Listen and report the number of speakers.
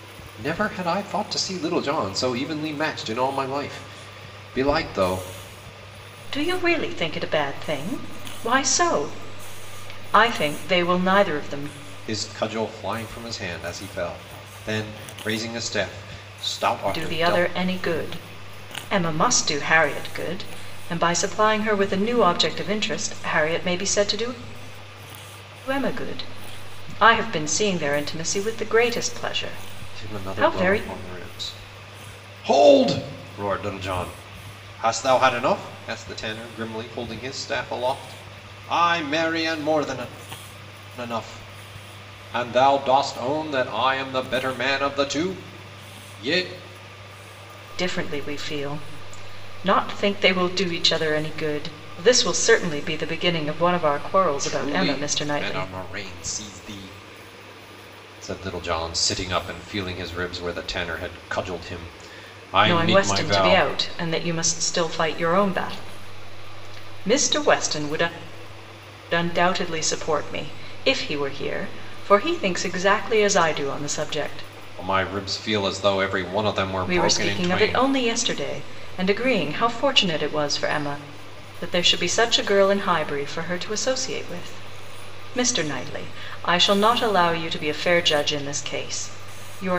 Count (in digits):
2